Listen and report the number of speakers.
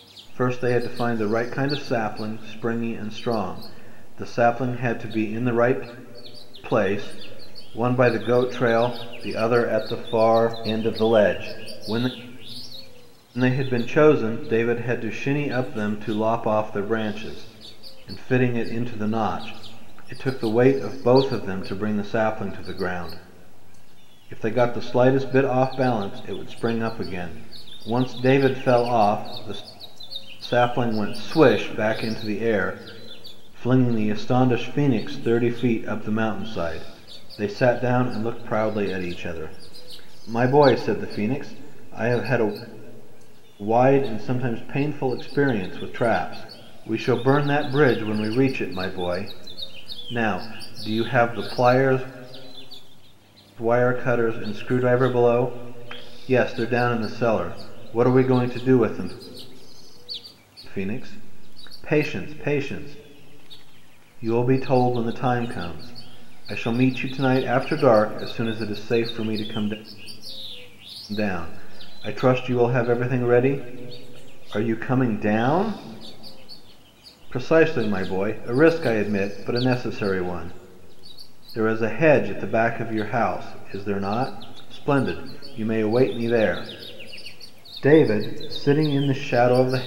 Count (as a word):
one